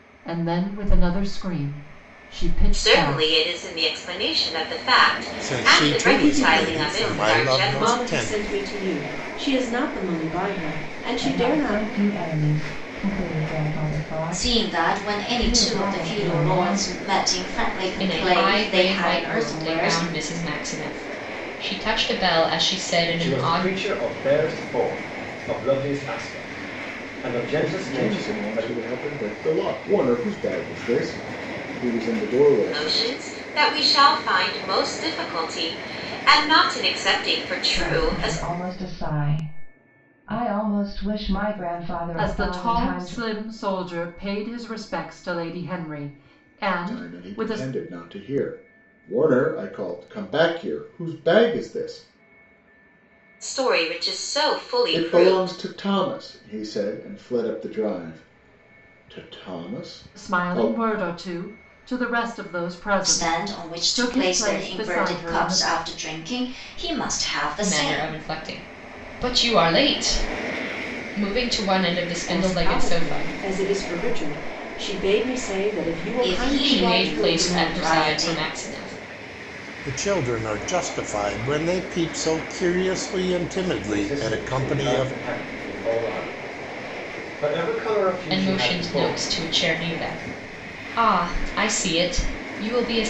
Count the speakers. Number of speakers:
9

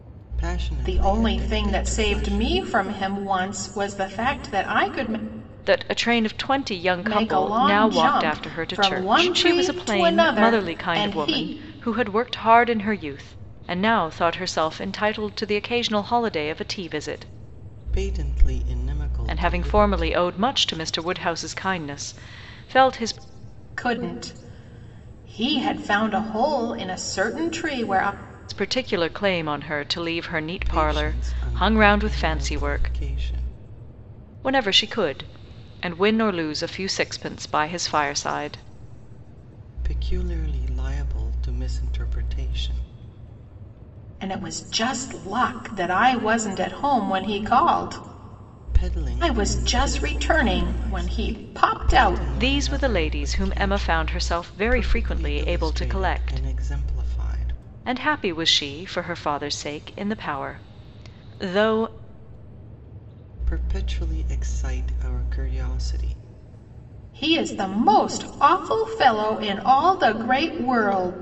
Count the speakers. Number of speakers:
3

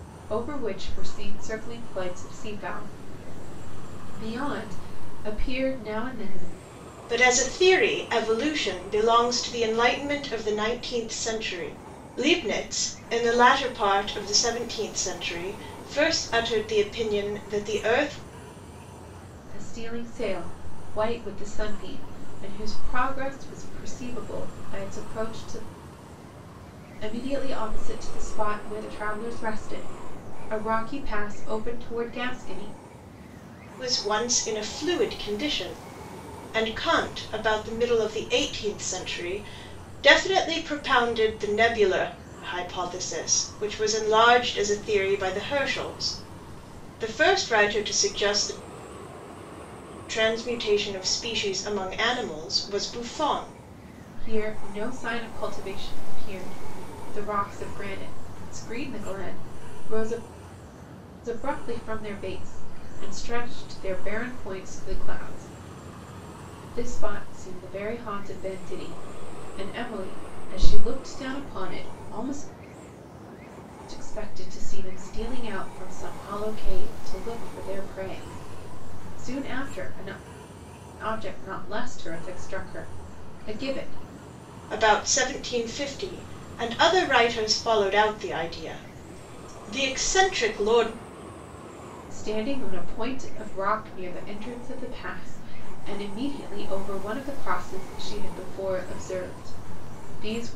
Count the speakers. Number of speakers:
2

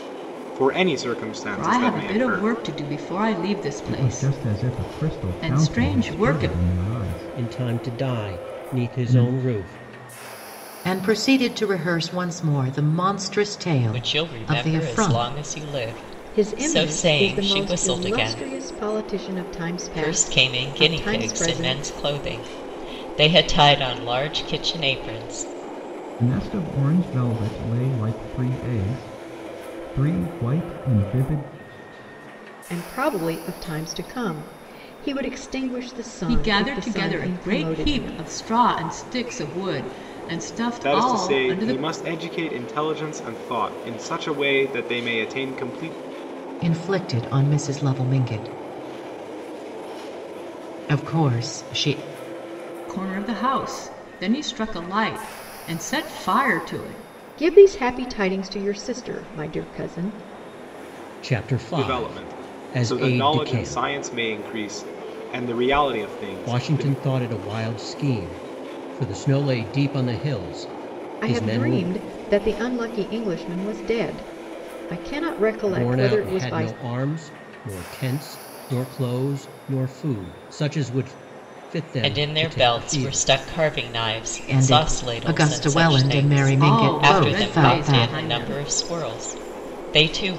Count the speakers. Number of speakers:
7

